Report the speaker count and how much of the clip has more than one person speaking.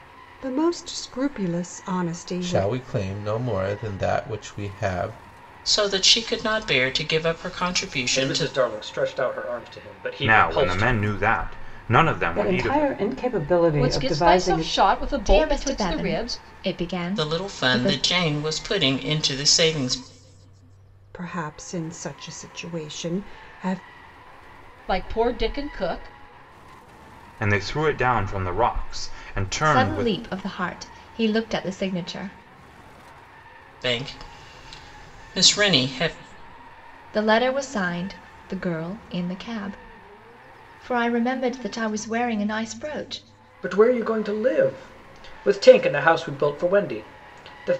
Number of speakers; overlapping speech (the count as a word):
eight, about 13%